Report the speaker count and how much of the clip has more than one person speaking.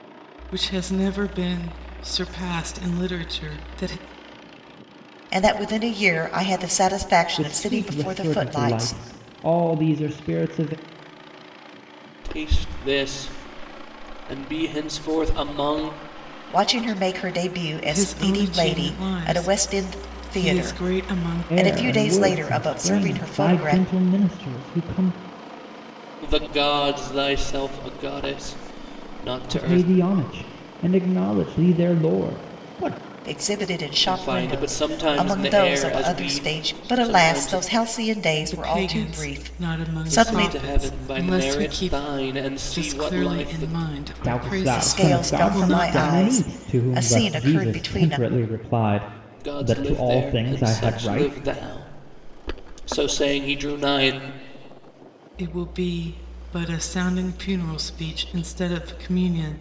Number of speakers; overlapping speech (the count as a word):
four, about 37%